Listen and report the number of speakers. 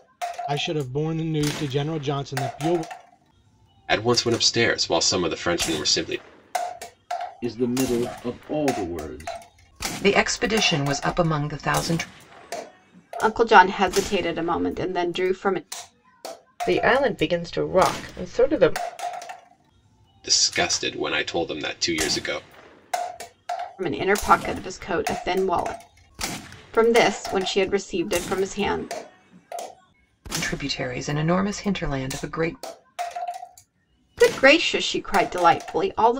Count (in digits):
6